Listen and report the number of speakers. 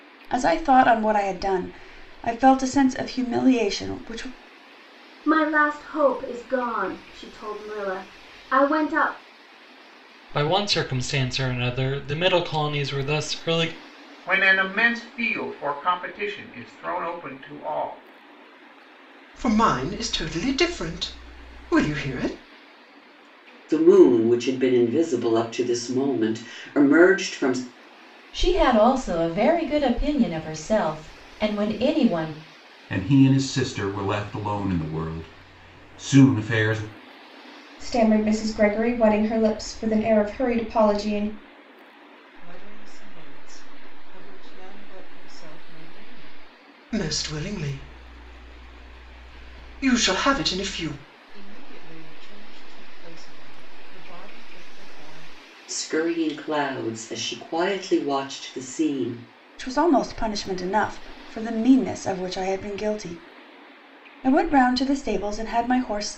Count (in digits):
10